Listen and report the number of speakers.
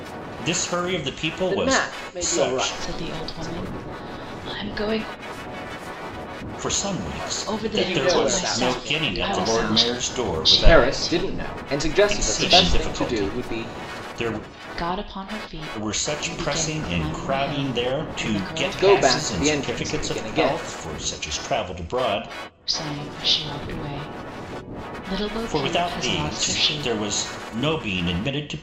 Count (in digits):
3